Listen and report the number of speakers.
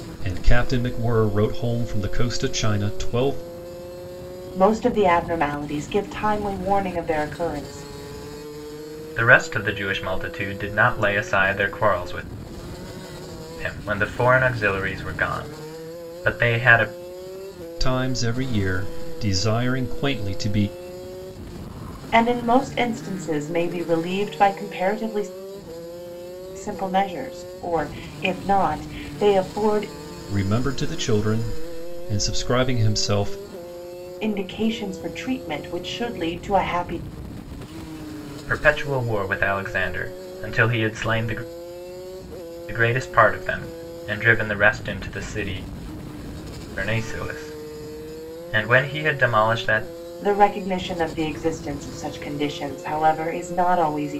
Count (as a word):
three